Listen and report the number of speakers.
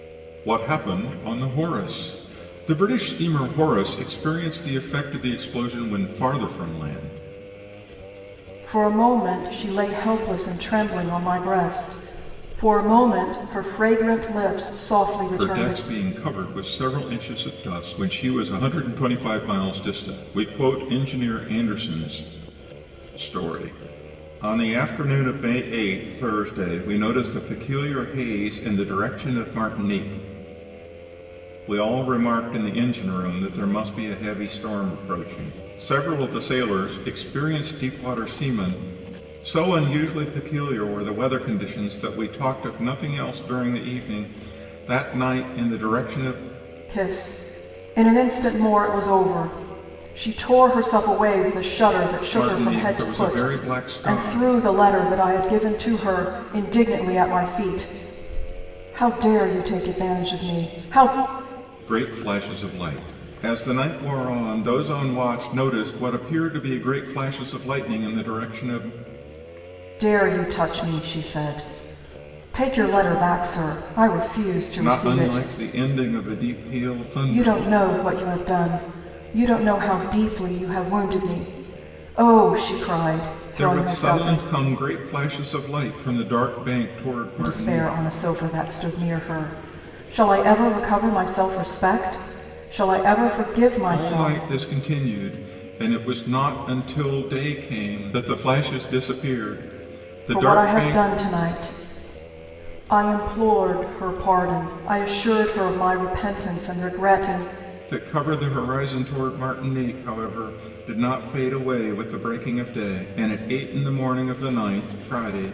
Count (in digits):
2